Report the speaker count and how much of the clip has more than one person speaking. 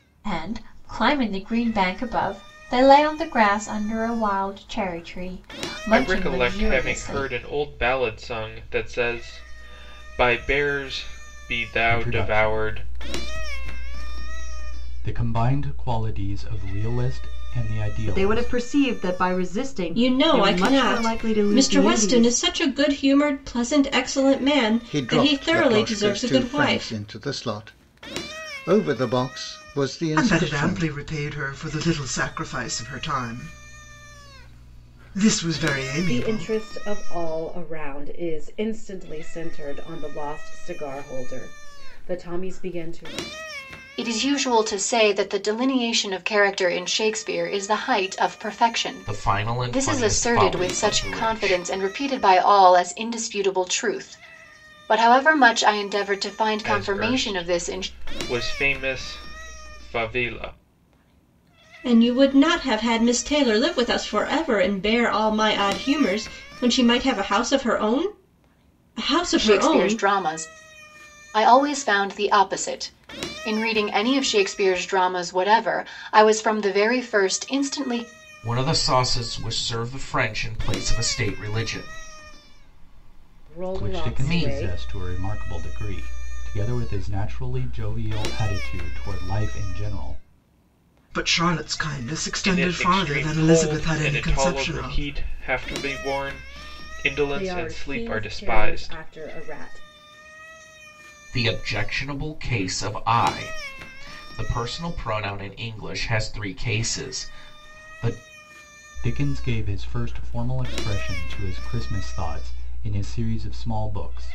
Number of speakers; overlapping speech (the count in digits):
10, about 17%